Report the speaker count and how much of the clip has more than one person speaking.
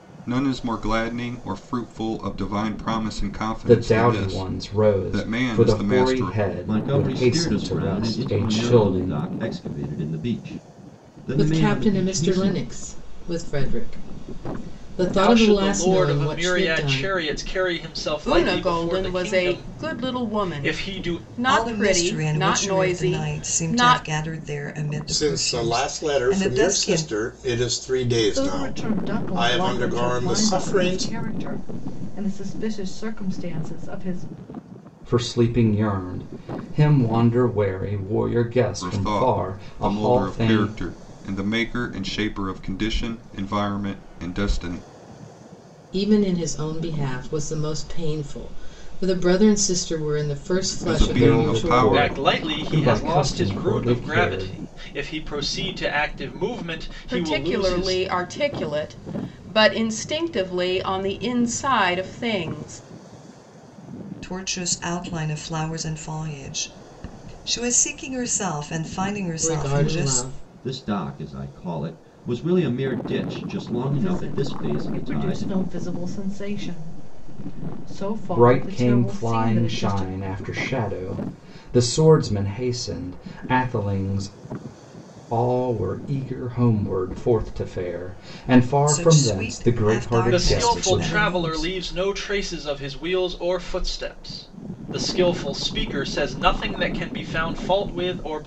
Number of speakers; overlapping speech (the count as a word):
nine, about 34%